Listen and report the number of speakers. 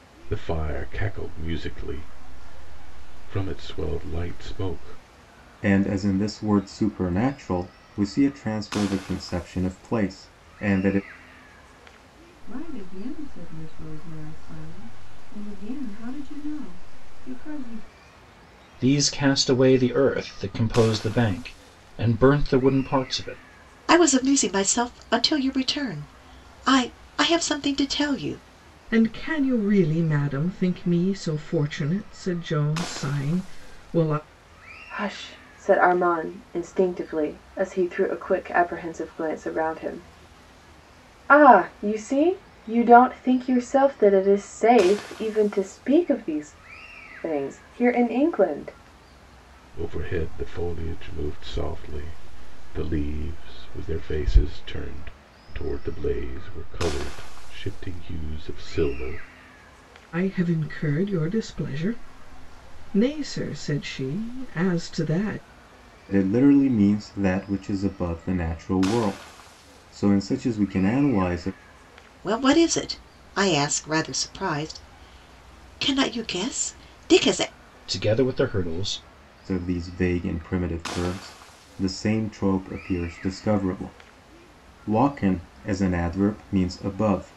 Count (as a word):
seven